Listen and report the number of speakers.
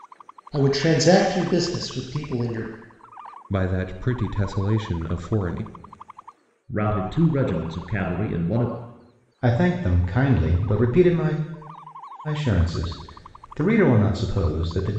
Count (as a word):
four